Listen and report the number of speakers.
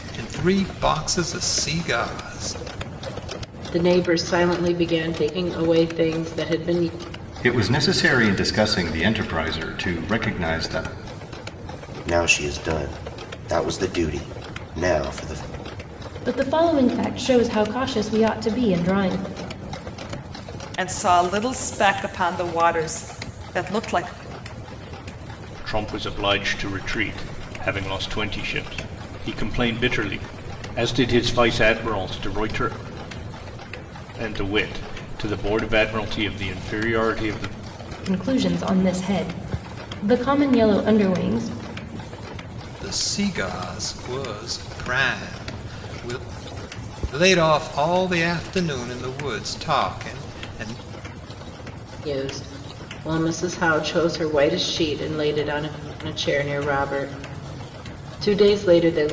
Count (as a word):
seven